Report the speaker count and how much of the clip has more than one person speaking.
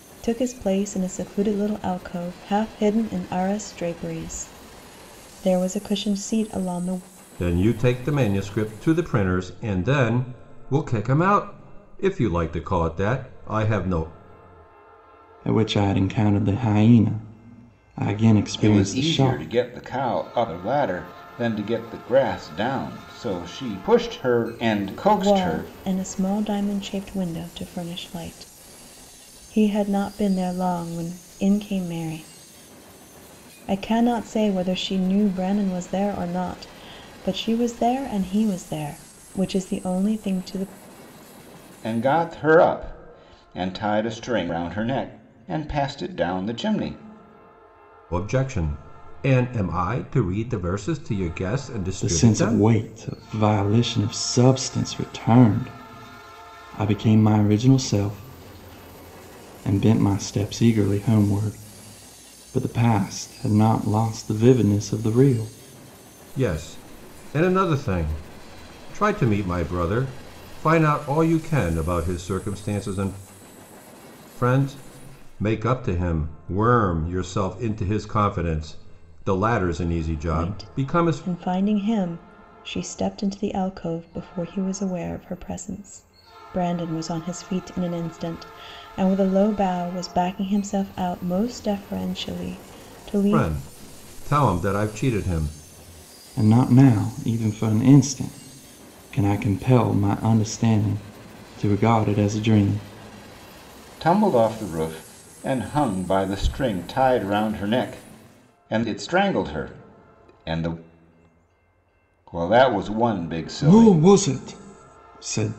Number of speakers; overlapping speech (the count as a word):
four, about 4%